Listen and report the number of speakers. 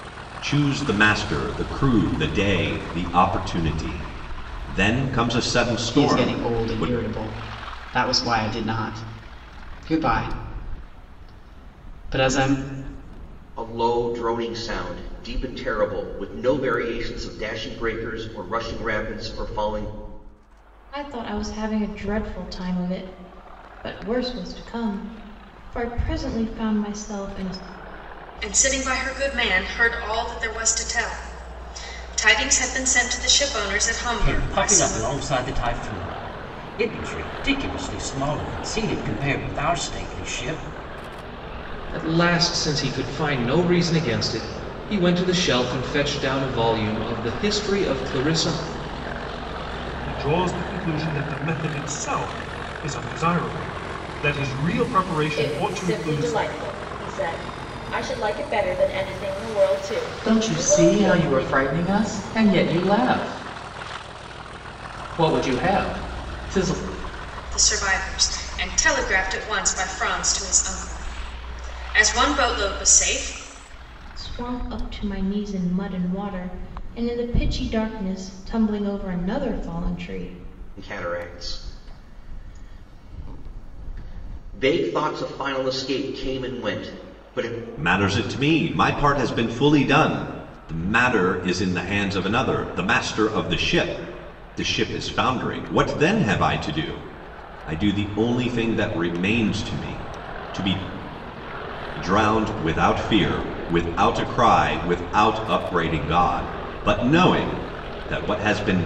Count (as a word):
ten